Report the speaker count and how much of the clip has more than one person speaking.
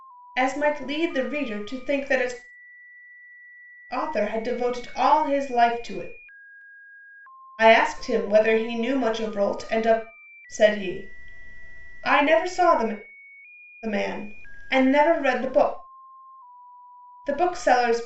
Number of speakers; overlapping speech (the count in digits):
1, no overlap